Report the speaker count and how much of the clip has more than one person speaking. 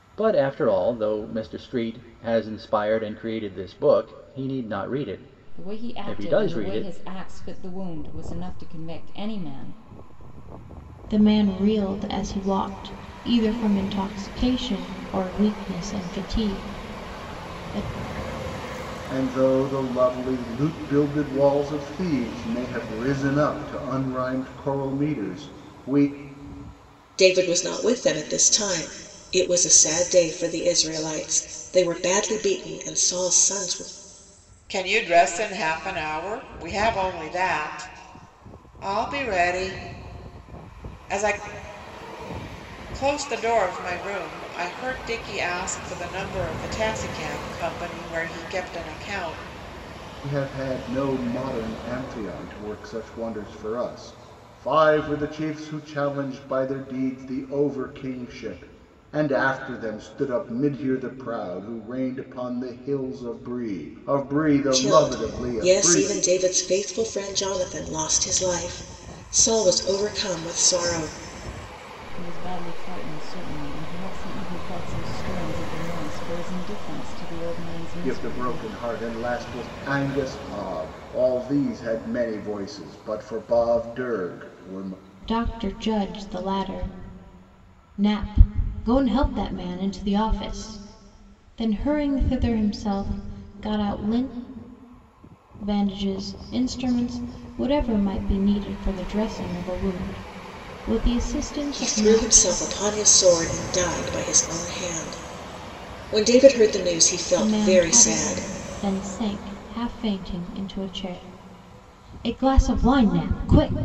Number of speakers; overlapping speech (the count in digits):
6, about 5%